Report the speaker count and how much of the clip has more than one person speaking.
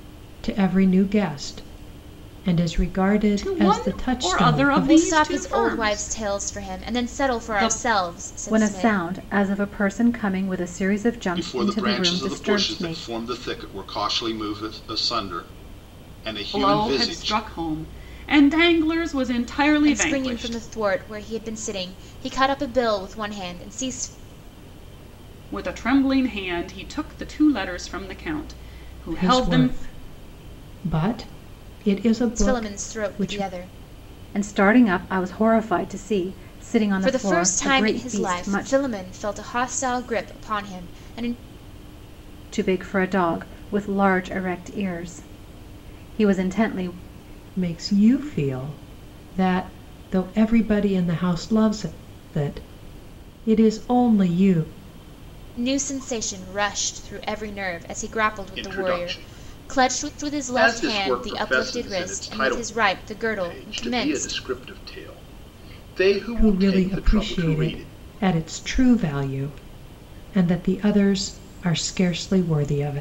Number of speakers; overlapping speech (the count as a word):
five, about 26%